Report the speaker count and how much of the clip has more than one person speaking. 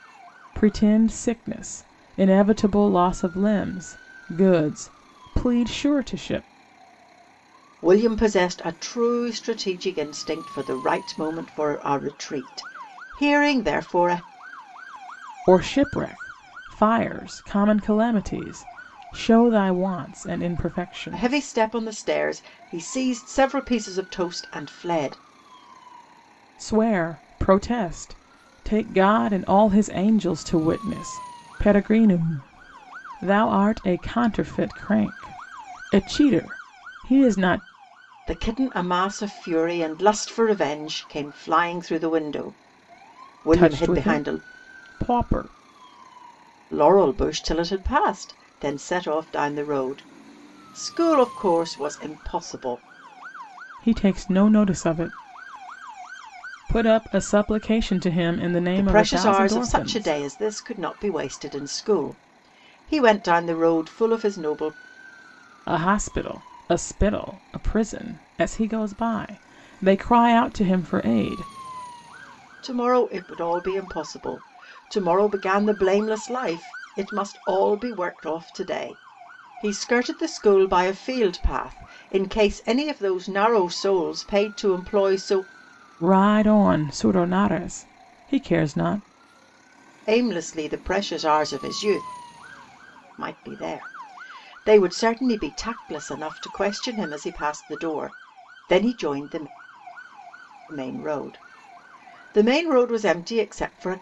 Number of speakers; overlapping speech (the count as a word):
two, about 3%